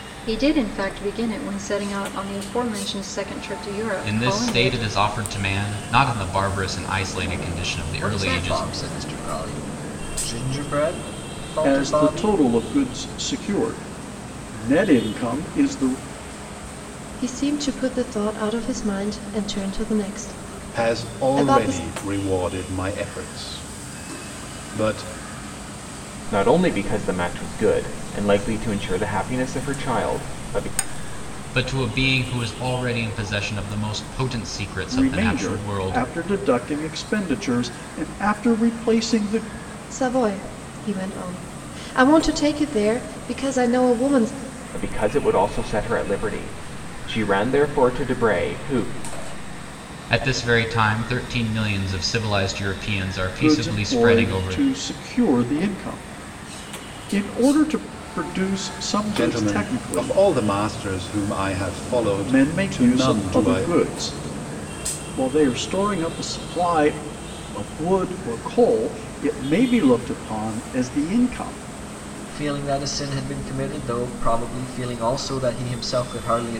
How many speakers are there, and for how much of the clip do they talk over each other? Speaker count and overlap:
seven, about 11%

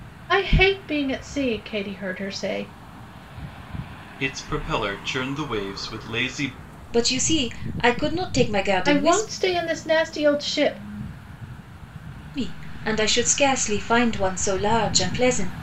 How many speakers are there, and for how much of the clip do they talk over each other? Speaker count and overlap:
three, about 3%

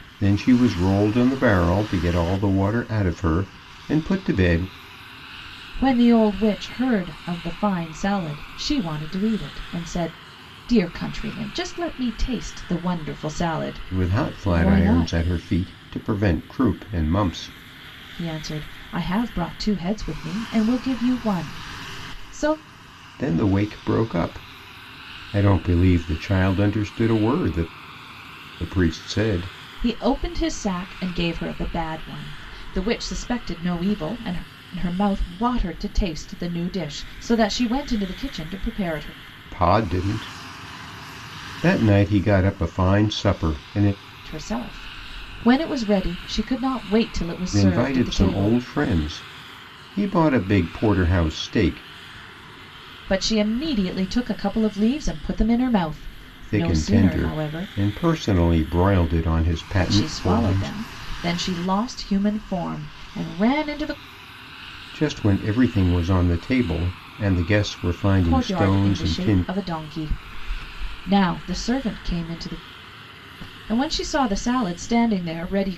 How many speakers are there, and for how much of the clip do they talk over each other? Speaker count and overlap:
two, about 8%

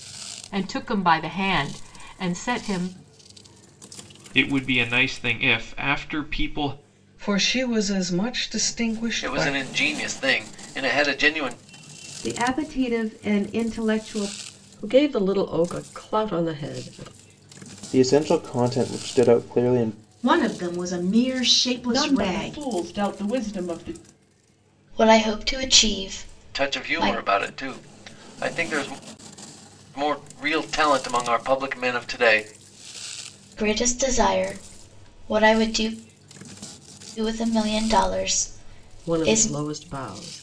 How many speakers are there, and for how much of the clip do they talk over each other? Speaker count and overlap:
ten, about 6%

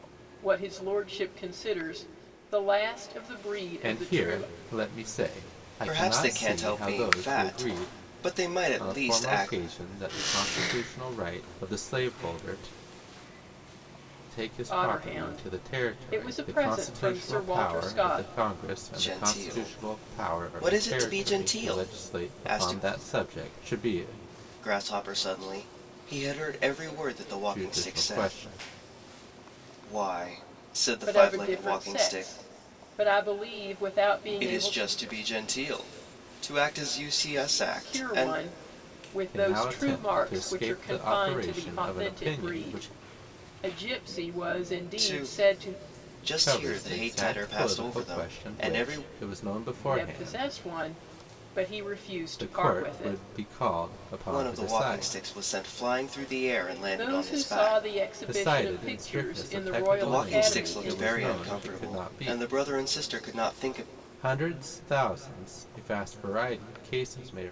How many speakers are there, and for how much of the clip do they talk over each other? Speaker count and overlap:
three, about 45%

